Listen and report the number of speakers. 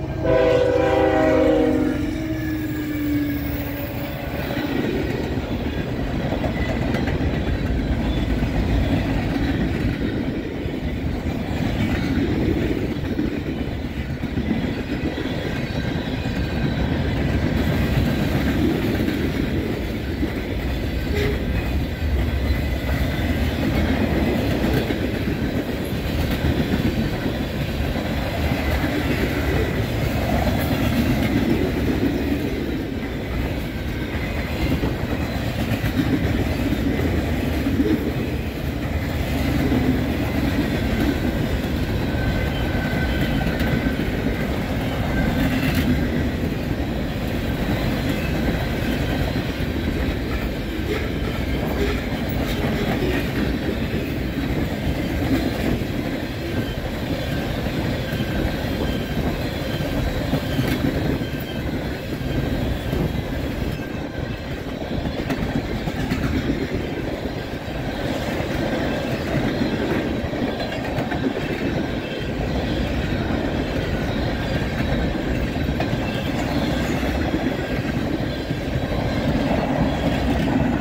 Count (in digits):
0